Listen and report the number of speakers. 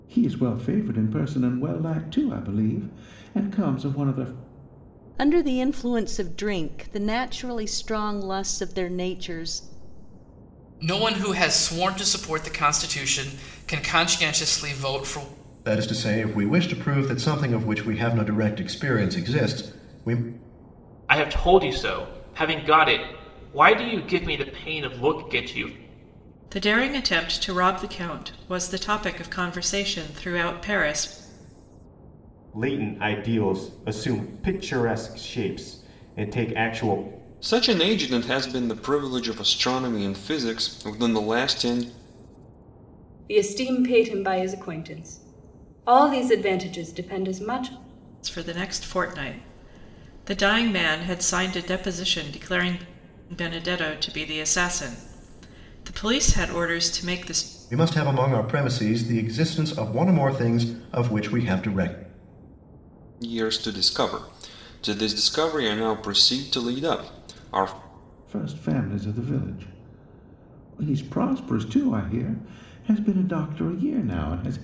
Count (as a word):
nine